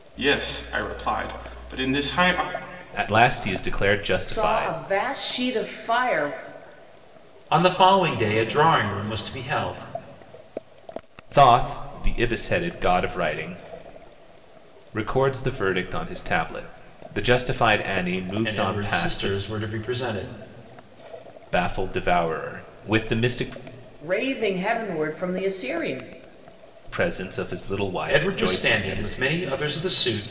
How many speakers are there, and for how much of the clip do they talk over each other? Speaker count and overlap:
four, about 9%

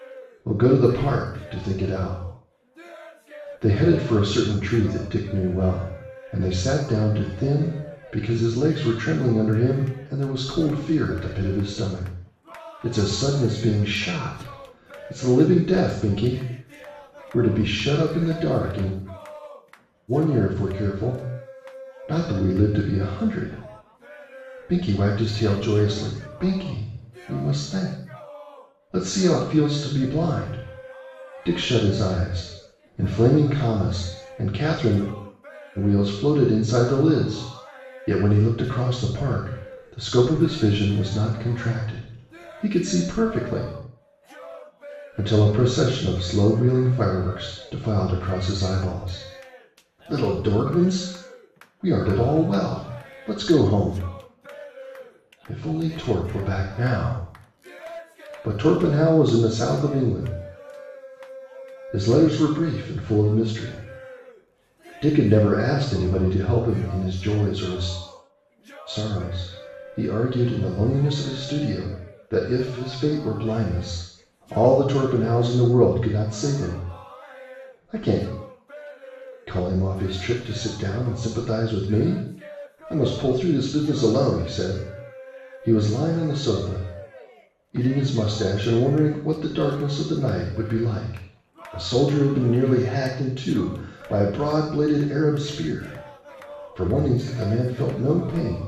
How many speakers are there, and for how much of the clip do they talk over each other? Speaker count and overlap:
one, no overlap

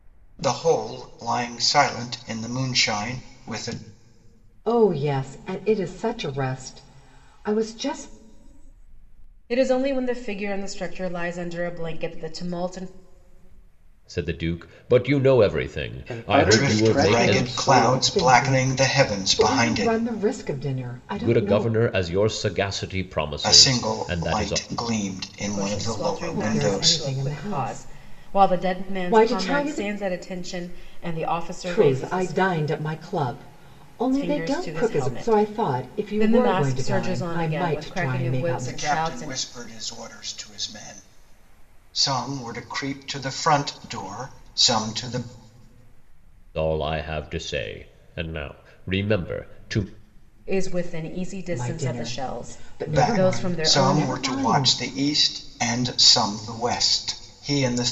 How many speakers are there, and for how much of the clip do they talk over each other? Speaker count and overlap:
five, about 33%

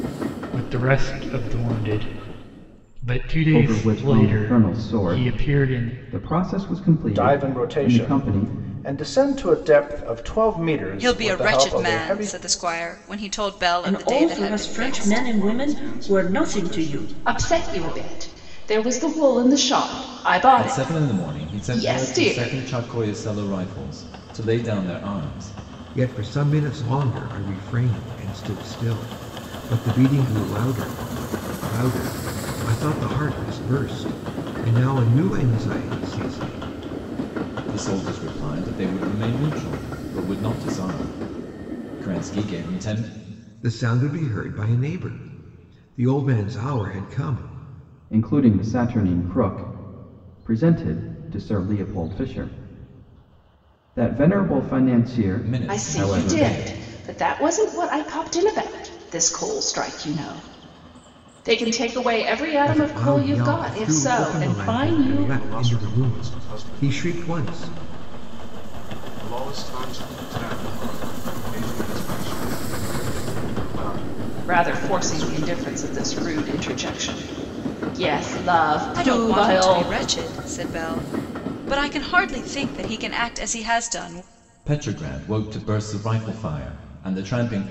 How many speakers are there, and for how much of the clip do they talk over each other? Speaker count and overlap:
nine, about 23%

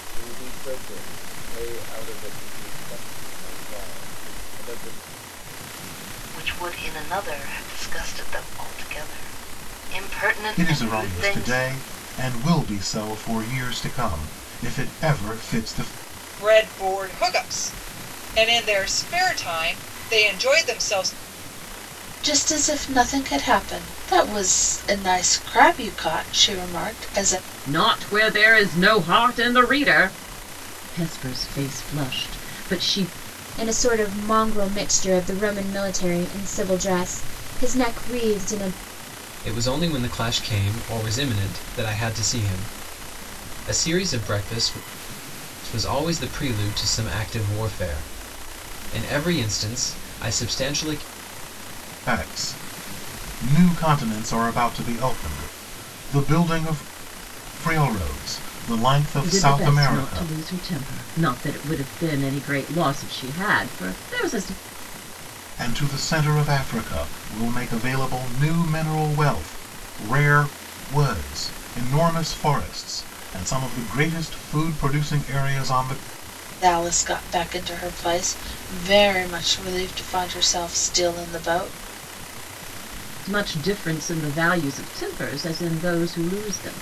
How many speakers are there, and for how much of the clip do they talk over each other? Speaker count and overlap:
eight, about 2%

